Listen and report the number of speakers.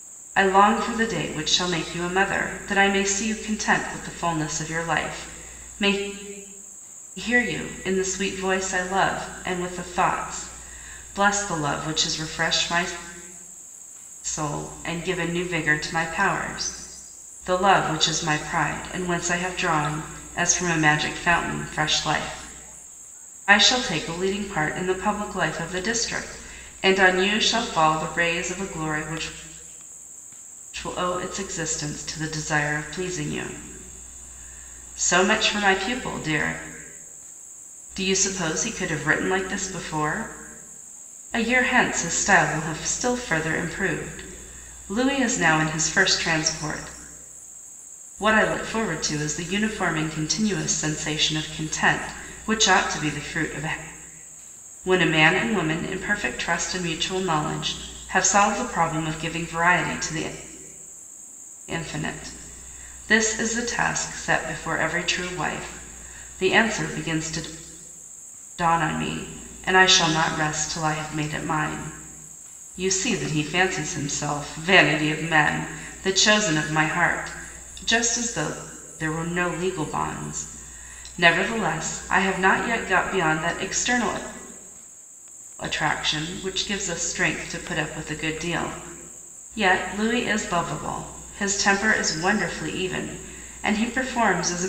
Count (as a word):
one